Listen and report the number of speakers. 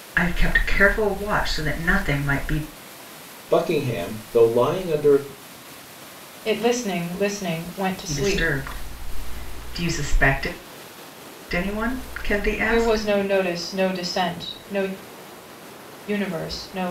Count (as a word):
three